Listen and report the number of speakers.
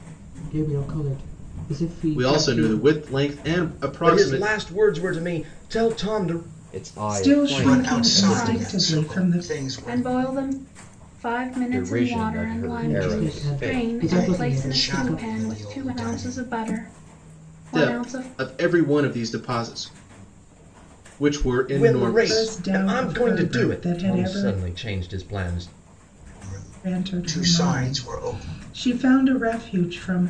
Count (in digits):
7